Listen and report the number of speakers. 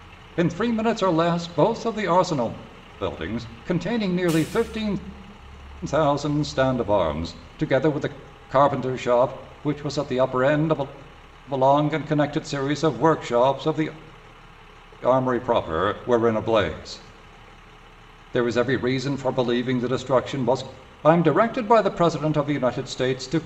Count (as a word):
one